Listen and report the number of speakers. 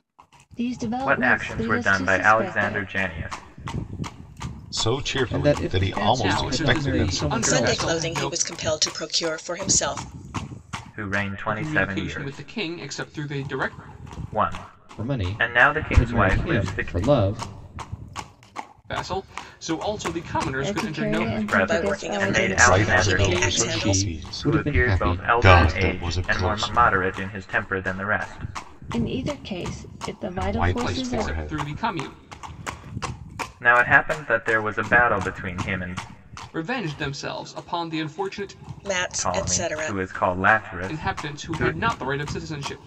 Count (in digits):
6